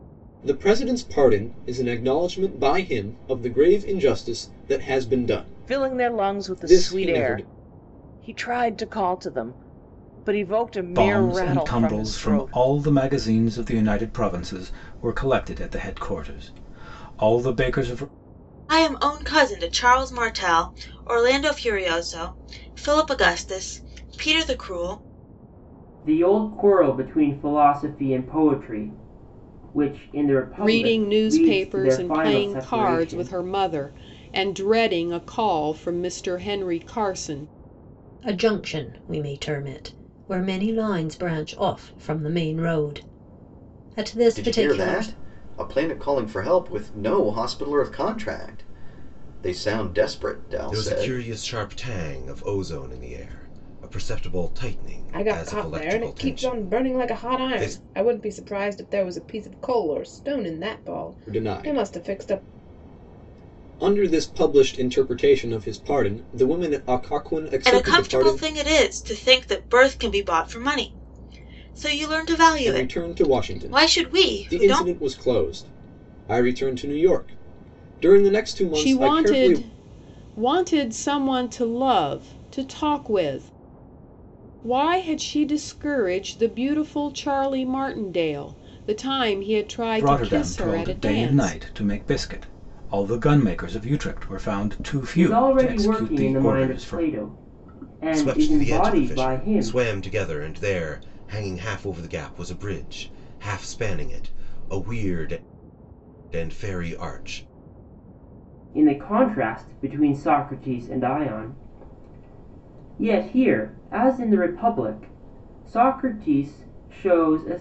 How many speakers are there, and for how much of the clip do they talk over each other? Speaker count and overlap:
ten, about 18%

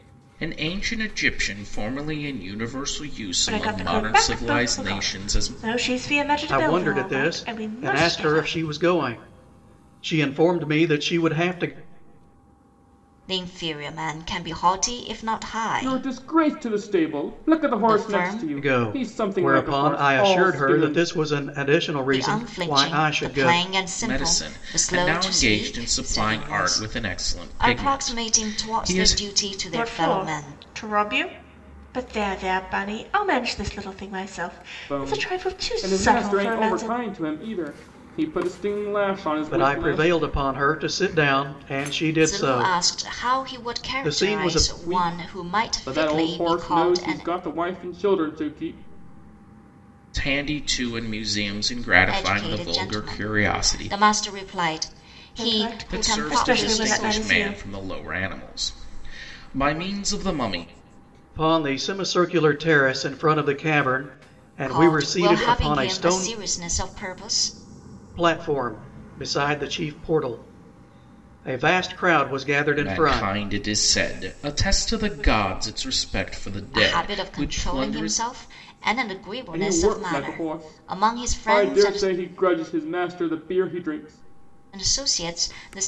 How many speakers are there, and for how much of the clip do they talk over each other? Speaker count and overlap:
five, about 40%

